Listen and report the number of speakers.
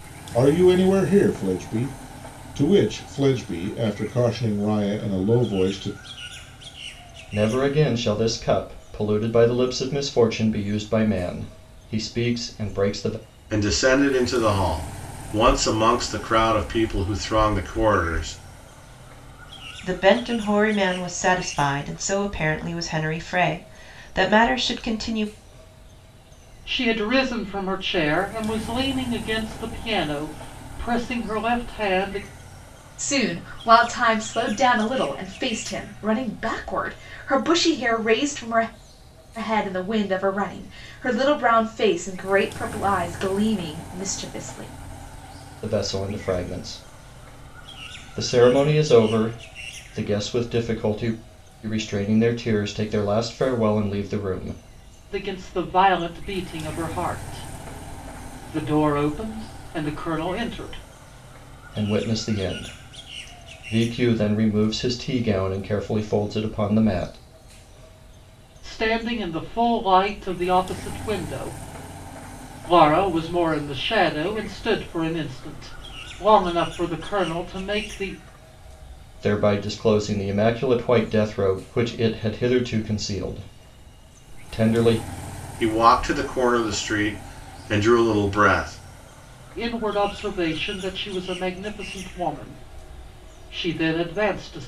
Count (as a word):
six